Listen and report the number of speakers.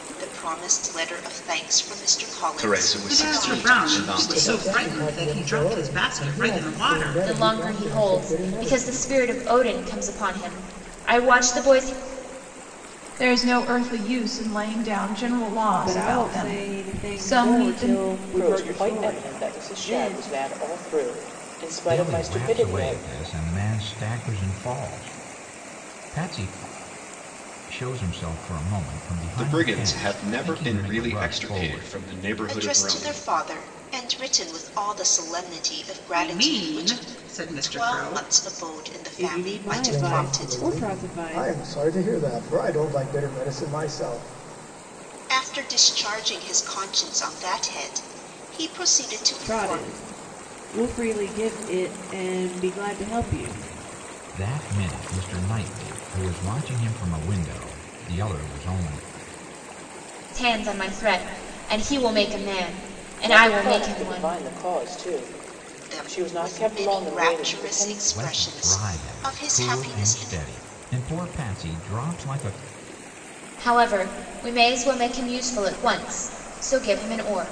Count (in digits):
9